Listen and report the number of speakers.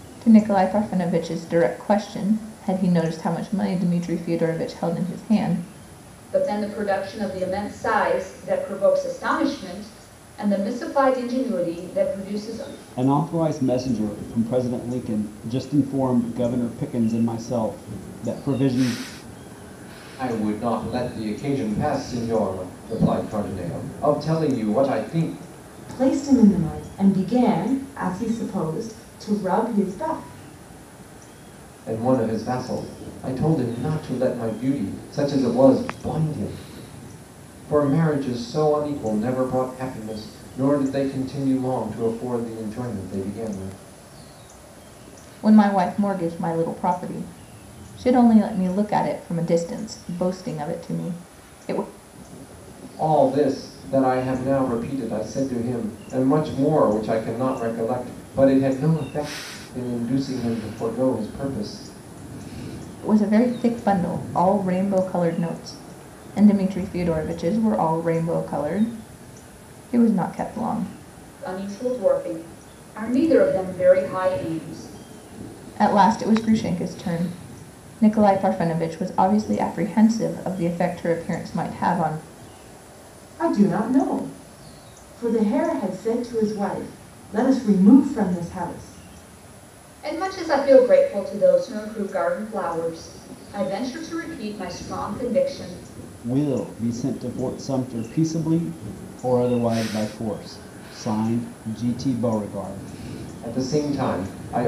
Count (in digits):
5